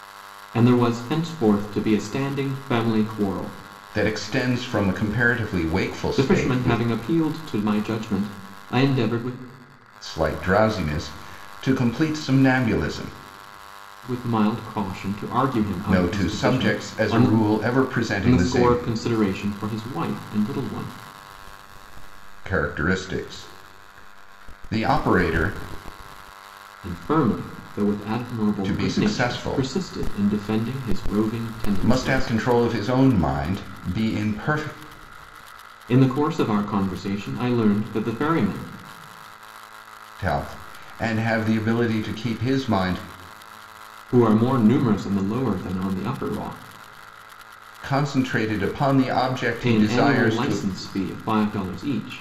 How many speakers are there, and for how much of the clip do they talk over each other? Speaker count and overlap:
2, about 11%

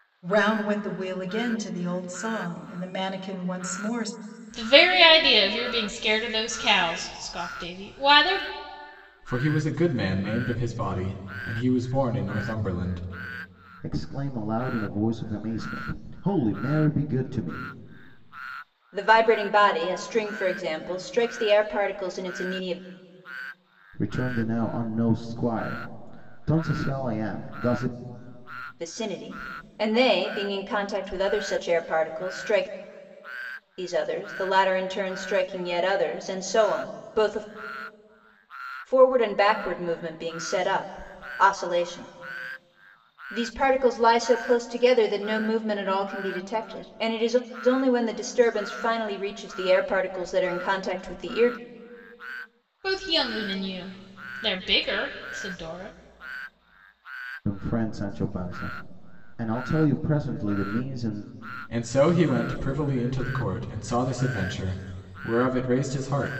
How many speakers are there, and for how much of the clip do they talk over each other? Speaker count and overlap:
5, no overlap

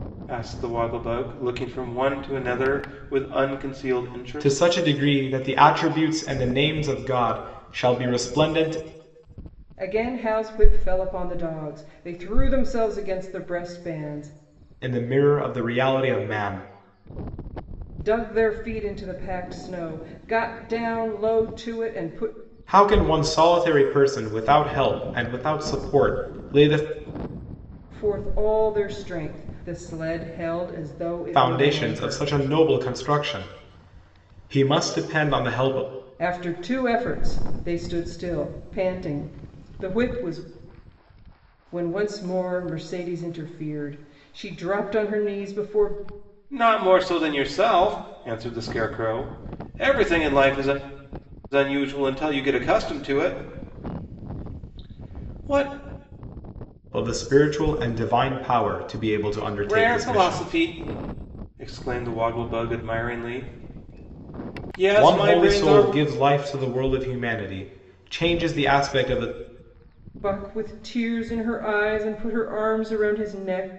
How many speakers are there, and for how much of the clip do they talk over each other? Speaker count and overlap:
3, about 4%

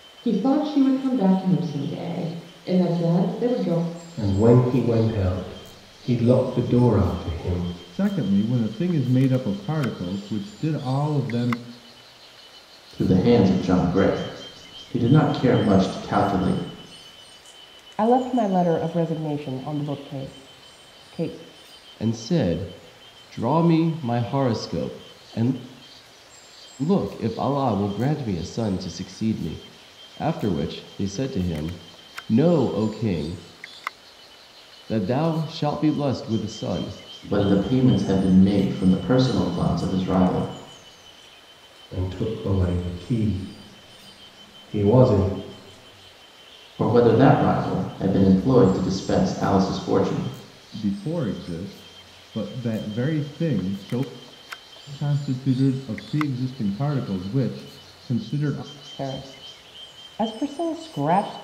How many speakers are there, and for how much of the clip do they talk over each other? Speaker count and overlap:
6, no overlap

